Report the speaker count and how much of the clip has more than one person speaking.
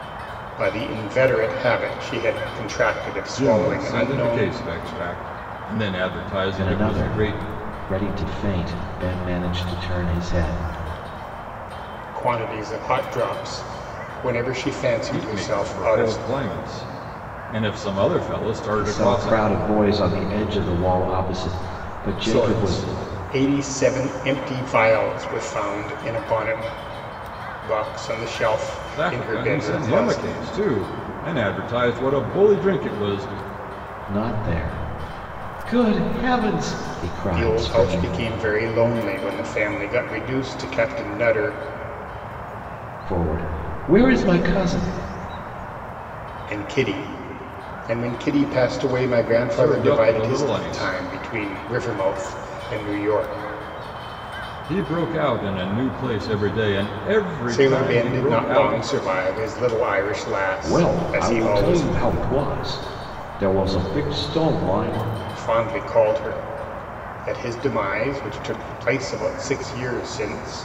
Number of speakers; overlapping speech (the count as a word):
three, about 15%